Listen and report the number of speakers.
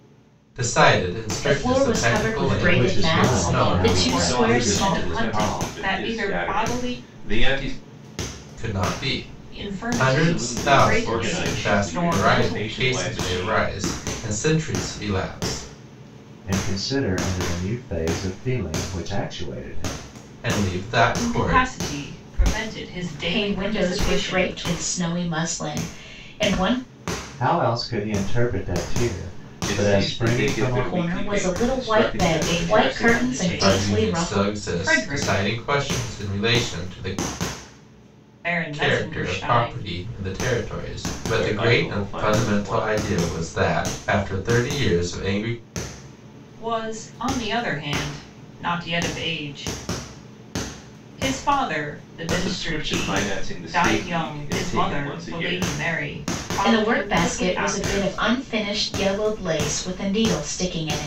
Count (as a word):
five